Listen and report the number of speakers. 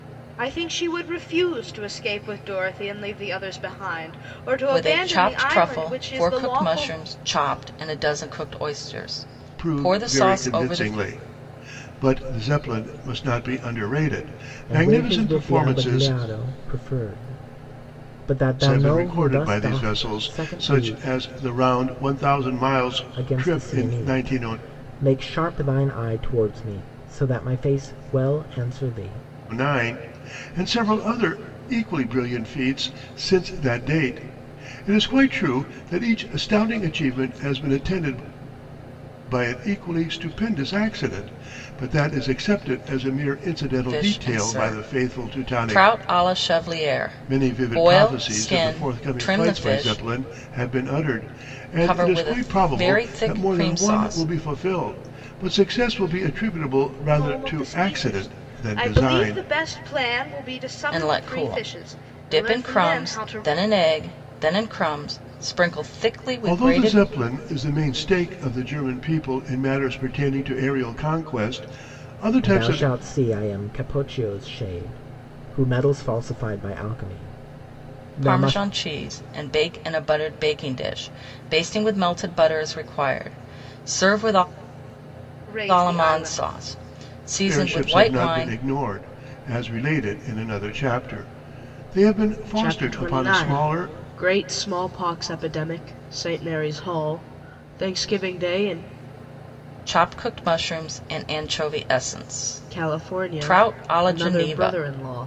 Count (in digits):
4